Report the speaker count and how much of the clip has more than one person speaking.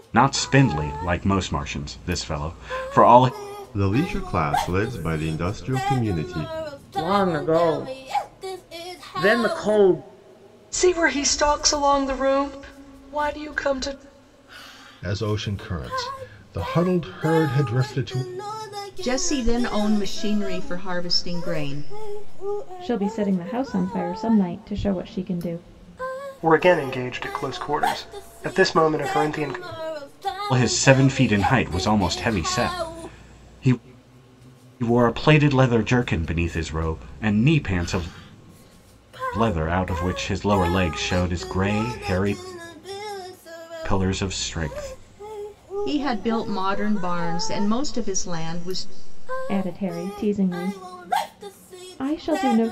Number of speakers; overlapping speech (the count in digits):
8, no overlap